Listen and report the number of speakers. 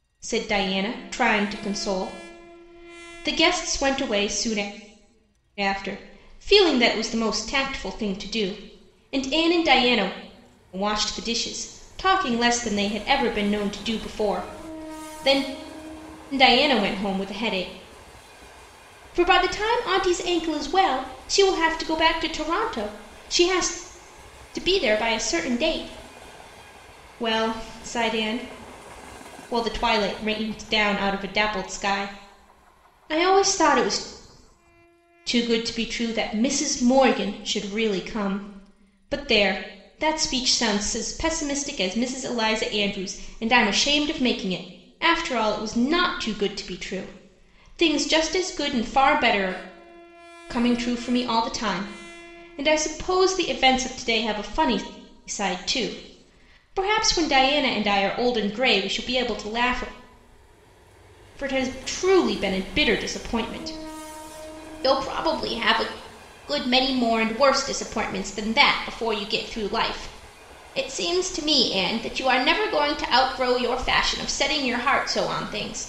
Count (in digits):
1